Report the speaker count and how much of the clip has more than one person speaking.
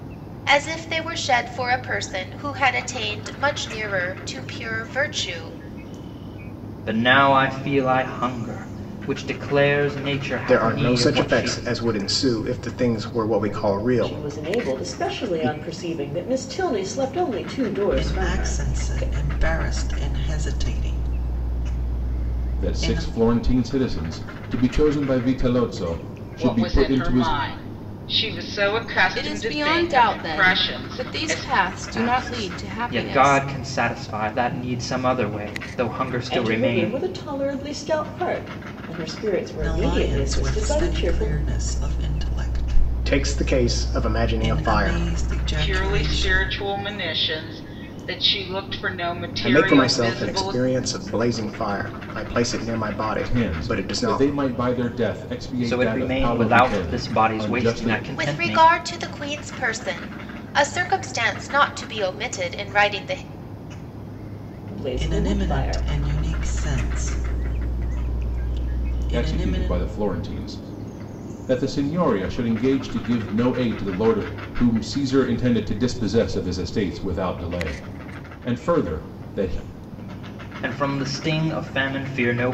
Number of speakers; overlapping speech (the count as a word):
eight, about 26%